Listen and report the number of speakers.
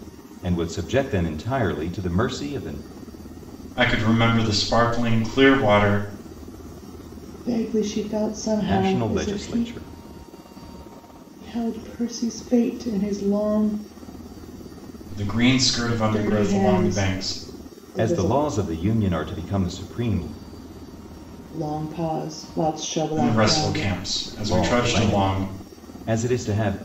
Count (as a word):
three